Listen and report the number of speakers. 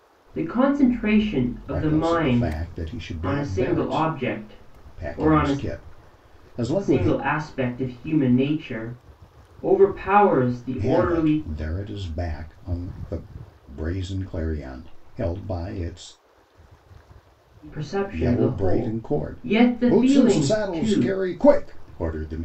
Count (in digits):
2